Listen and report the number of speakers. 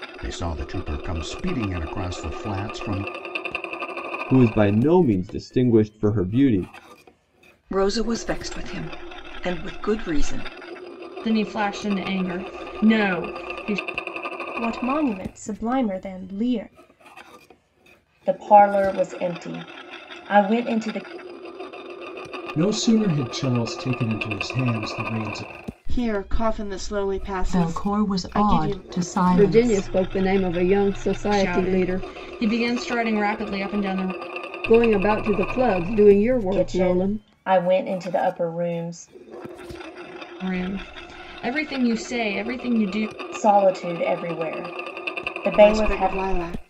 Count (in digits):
10